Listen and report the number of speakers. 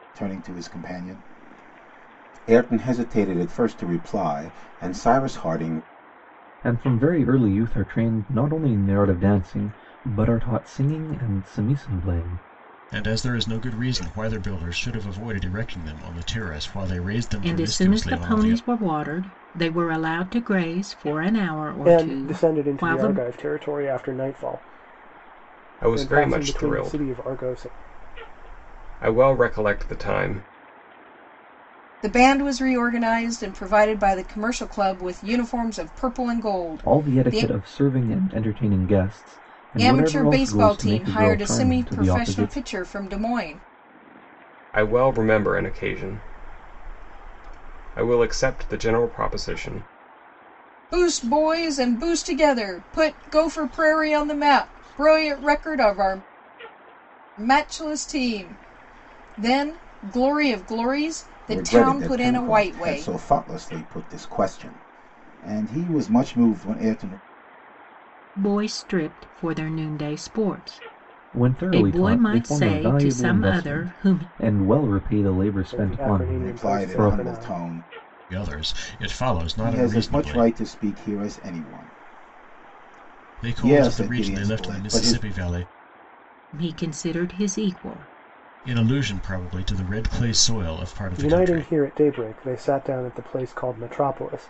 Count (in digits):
7